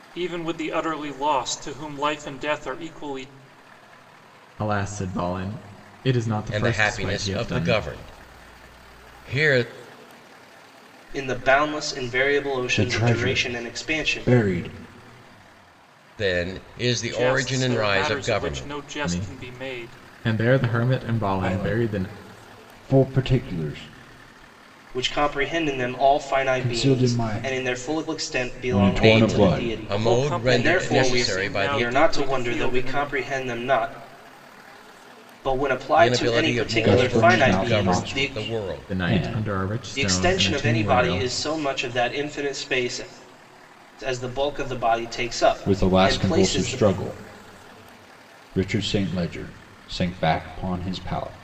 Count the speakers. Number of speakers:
5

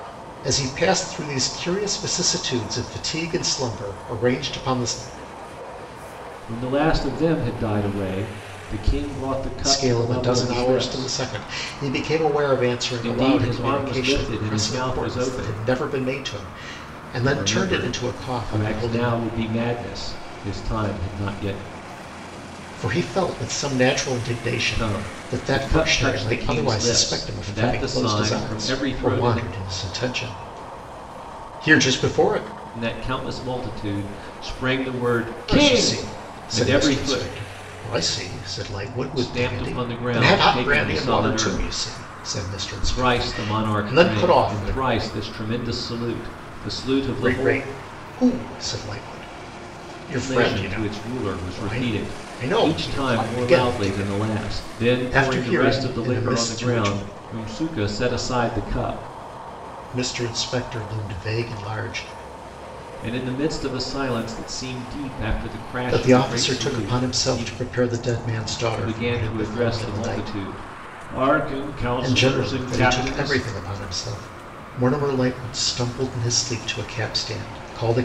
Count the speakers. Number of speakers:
2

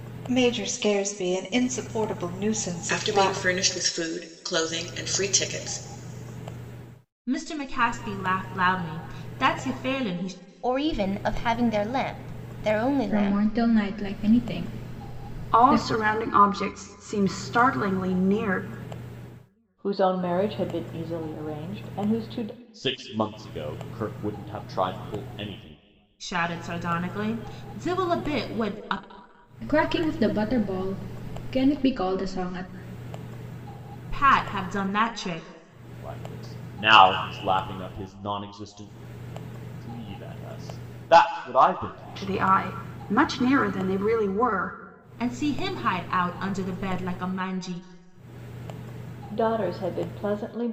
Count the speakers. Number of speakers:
8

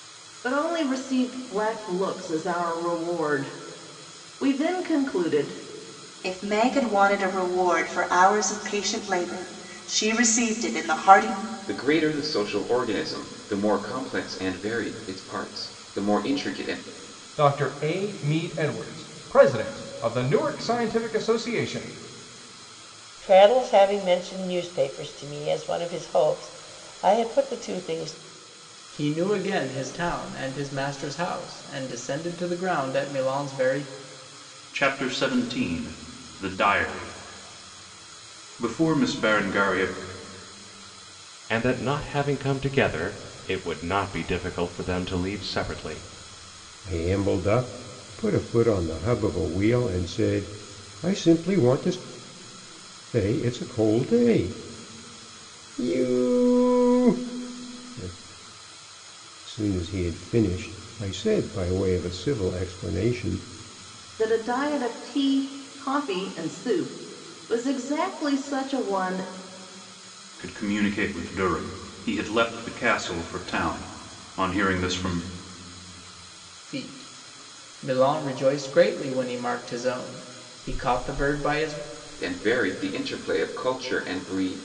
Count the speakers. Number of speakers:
9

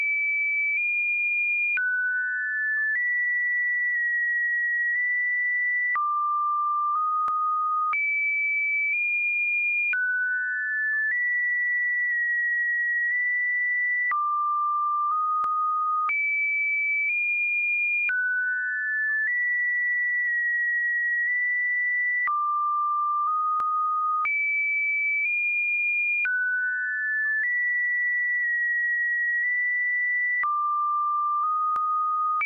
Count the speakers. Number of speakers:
0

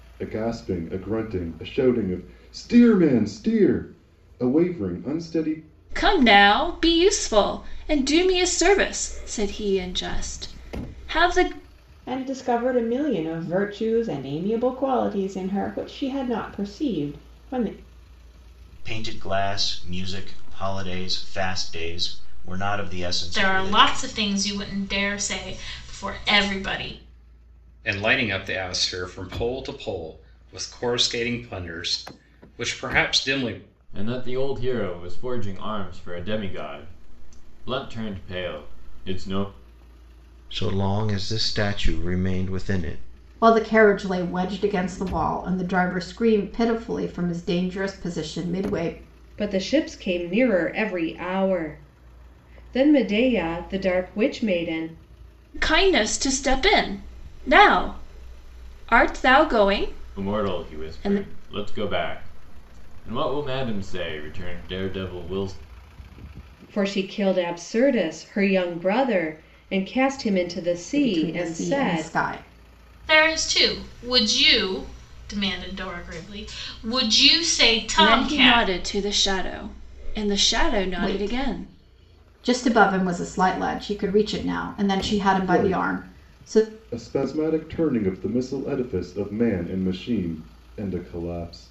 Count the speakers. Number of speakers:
10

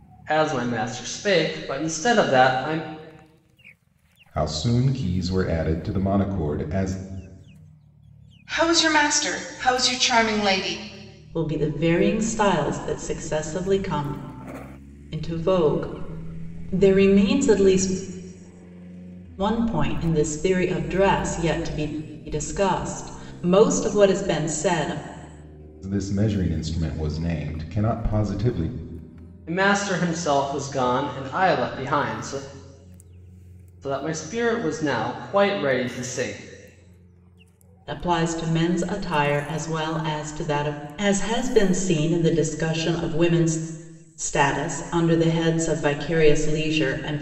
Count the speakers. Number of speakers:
4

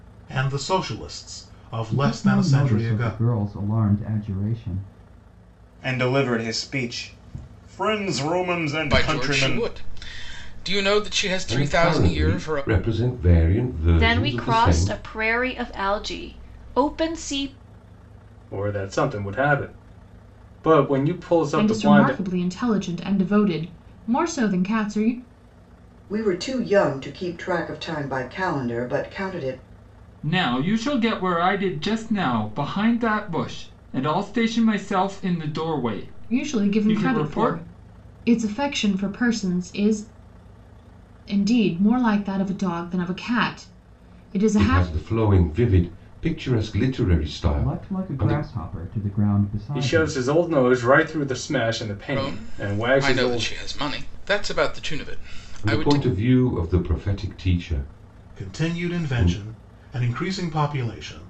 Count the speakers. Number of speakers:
10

